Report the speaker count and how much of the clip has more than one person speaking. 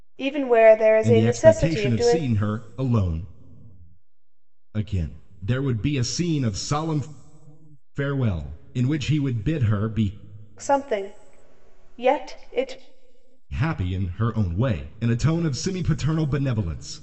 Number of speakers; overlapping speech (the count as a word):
two, about 8%